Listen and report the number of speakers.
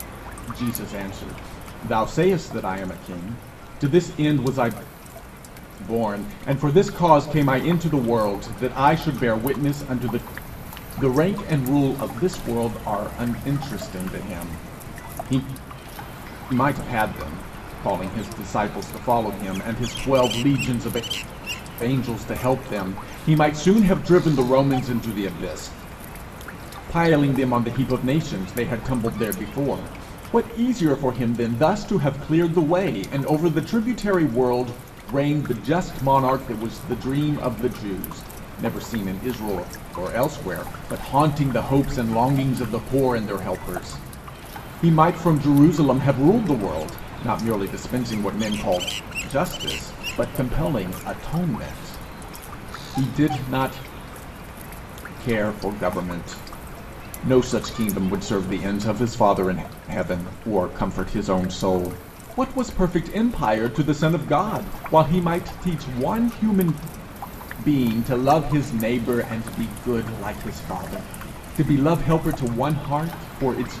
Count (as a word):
one